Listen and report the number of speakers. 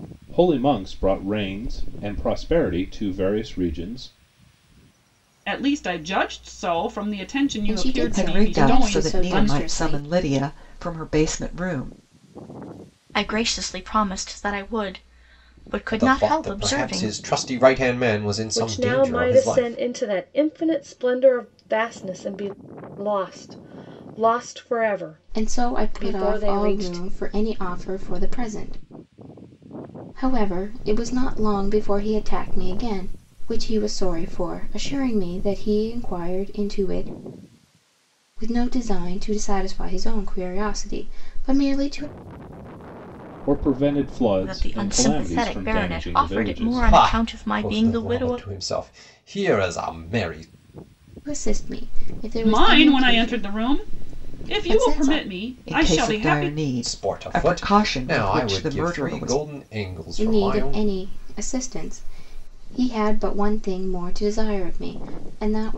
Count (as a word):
seven